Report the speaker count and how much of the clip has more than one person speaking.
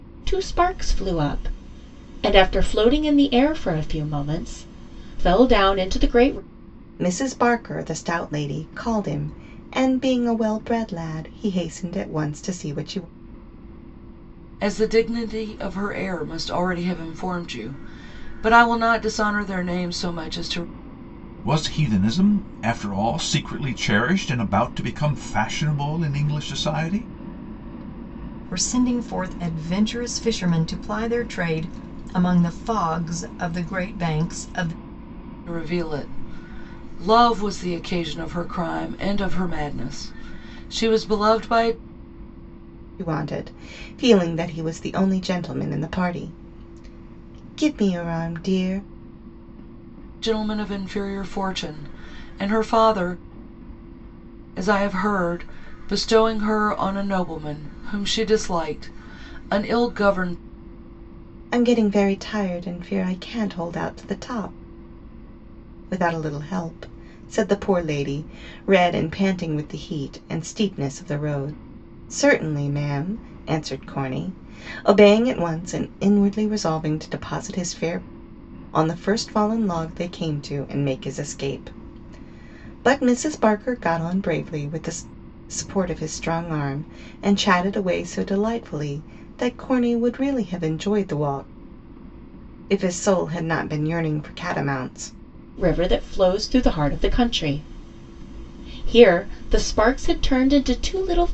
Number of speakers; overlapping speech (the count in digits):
5, no overlap